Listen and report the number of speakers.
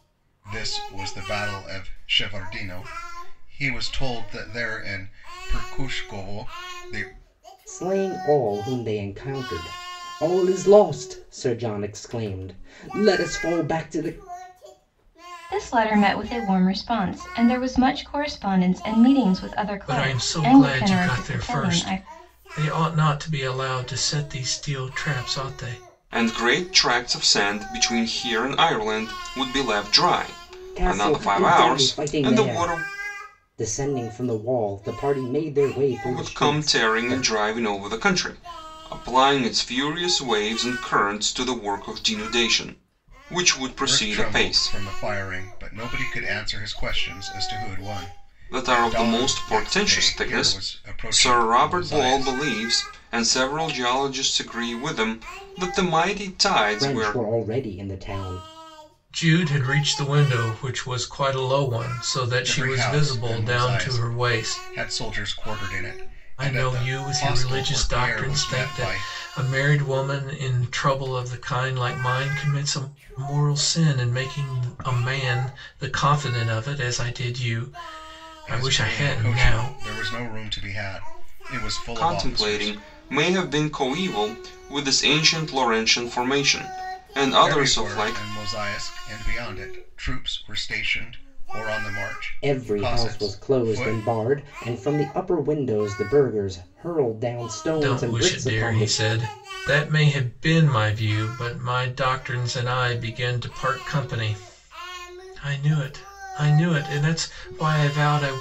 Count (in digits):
5